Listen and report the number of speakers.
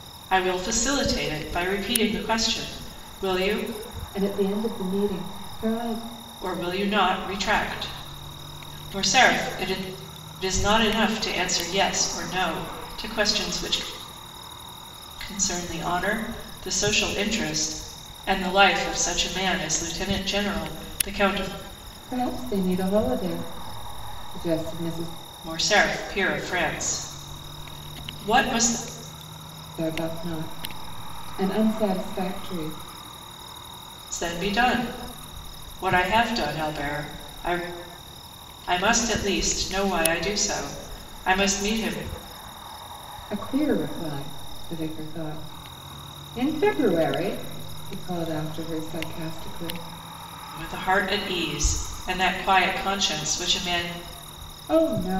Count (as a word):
two